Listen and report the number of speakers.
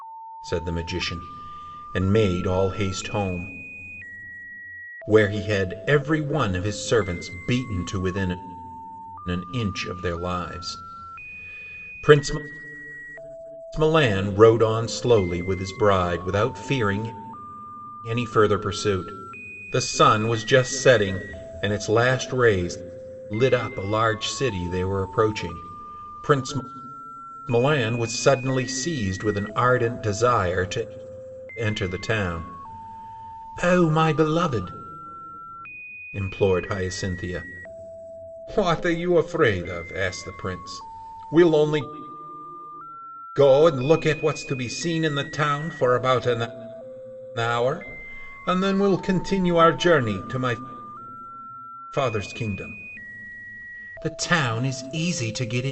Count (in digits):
1